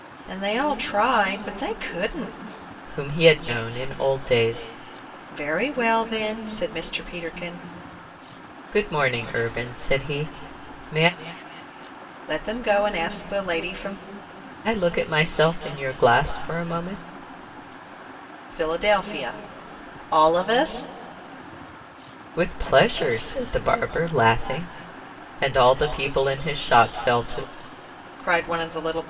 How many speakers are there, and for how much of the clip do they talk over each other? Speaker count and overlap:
2, no overlap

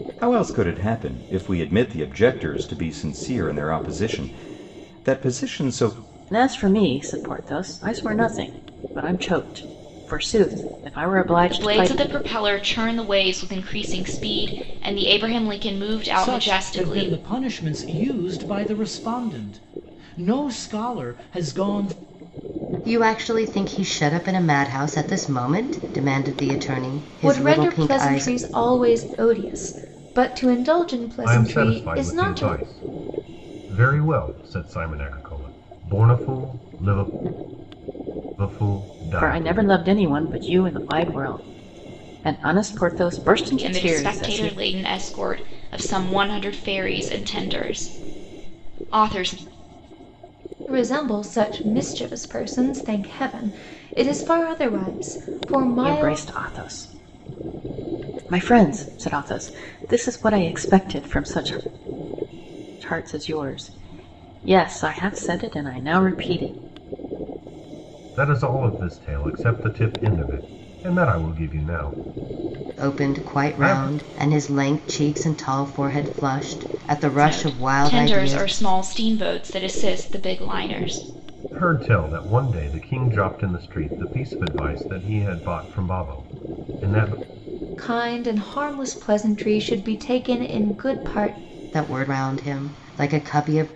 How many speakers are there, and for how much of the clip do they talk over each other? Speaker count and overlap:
7, about 9%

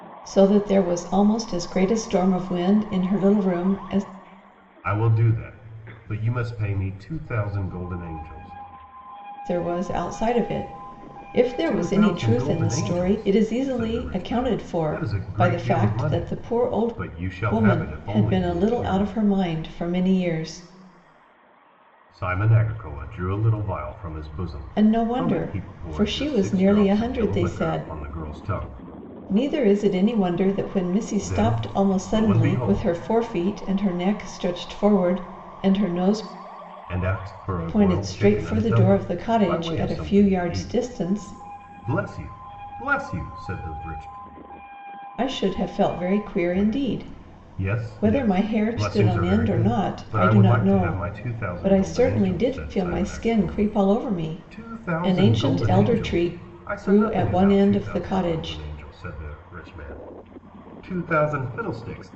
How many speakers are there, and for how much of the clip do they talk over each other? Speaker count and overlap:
2, about 43%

